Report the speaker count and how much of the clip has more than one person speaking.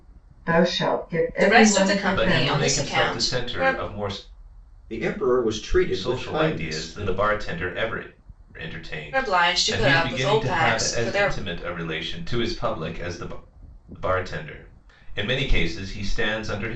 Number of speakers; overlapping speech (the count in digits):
4, about 35%